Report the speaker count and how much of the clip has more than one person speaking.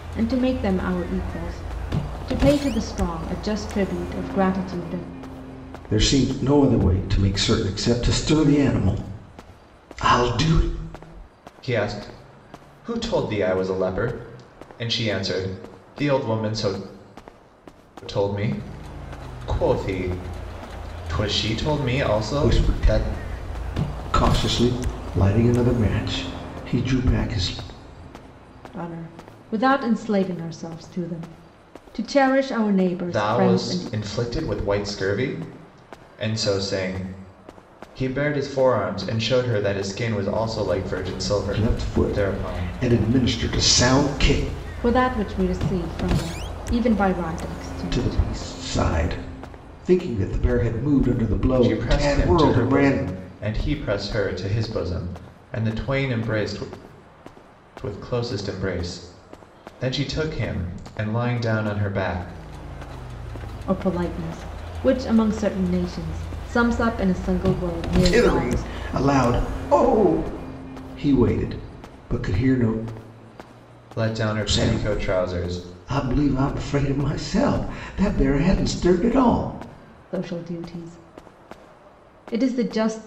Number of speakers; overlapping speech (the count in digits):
3, about 9%